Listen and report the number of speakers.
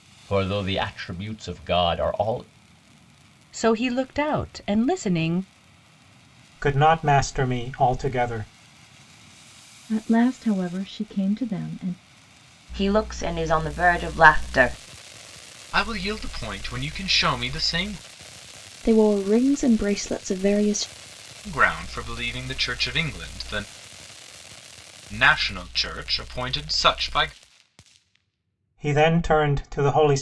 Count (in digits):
7